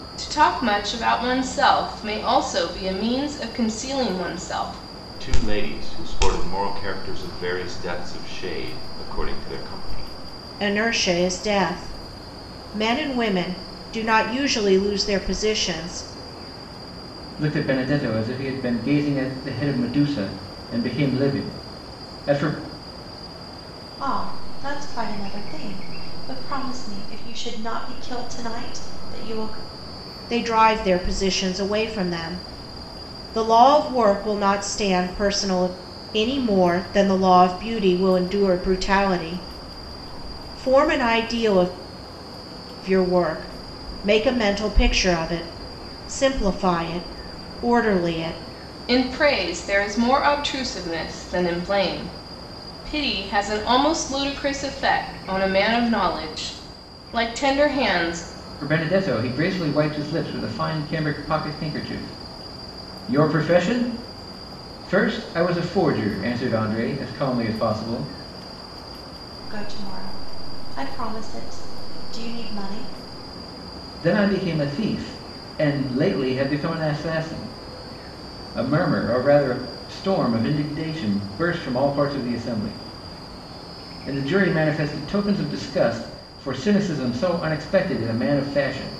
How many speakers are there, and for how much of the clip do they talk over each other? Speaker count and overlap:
five, no overlap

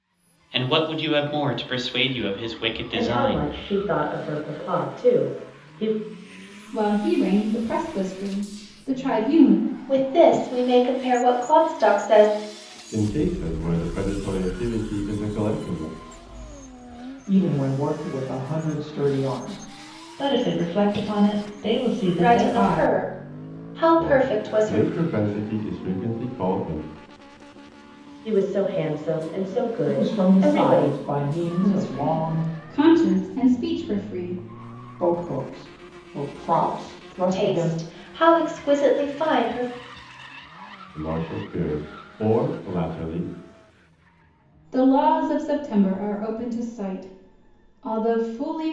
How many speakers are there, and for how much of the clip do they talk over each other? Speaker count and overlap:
seven, about 10%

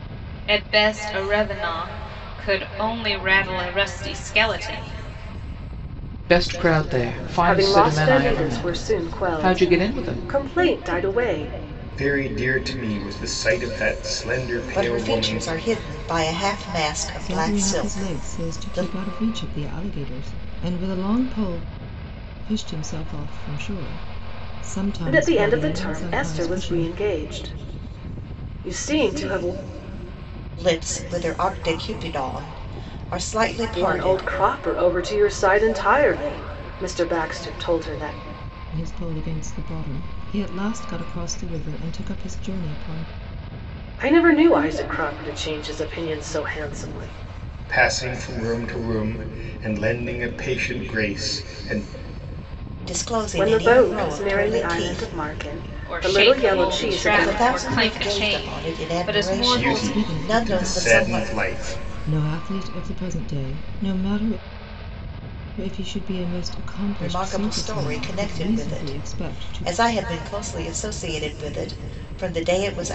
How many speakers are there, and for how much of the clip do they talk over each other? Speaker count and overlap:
six, about 25%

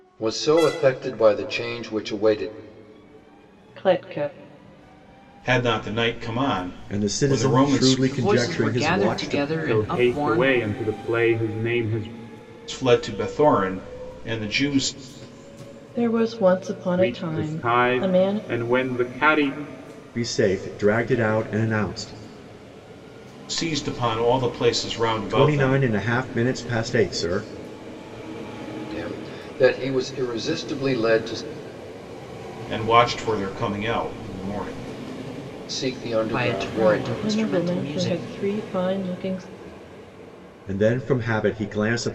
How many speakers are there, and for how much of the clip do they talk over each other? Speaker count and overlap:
six, about 18%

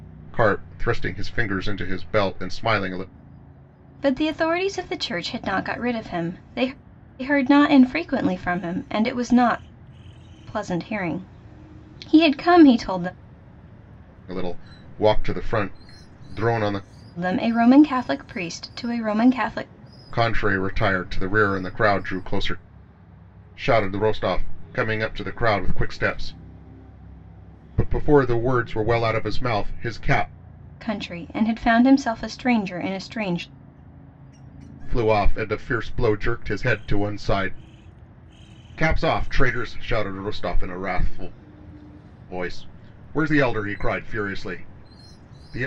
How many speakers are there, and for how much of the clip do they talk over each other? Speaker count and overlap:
two, no overlap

